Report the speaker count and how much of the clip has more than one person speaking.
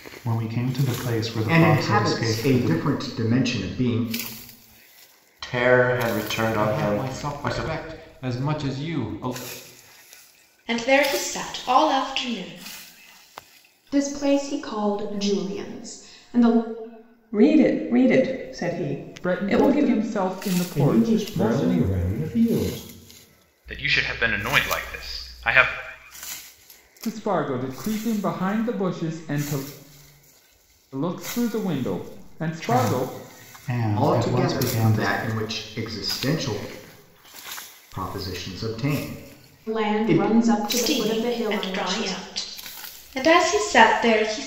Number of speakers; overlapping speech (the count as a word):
ten, about 19%